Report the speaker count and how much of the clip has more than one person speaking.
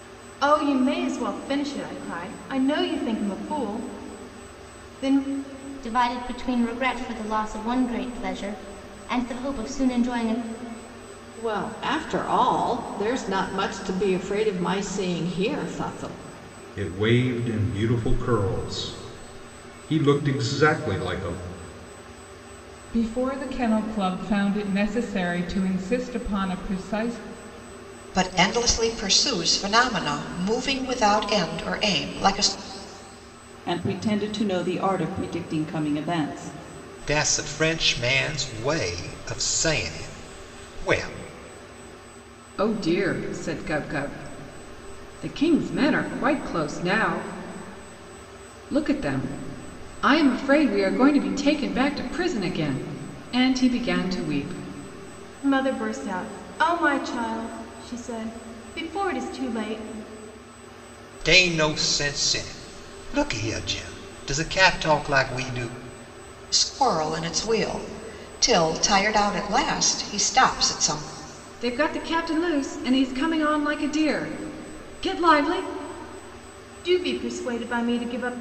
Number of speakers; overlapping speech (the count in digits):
9, no overlap